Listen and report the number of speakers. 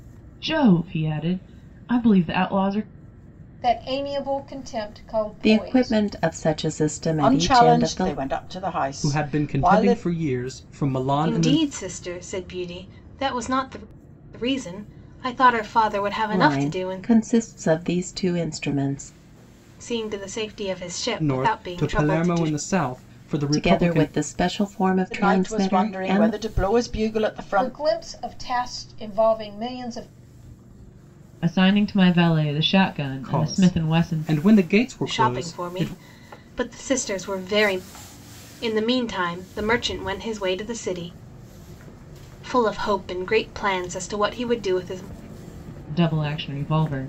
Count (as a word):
six